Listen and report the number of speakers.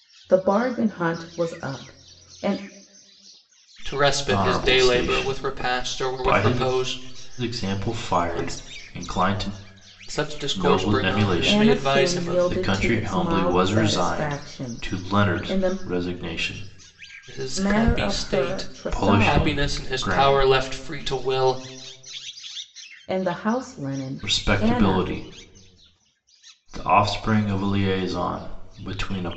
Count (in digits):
3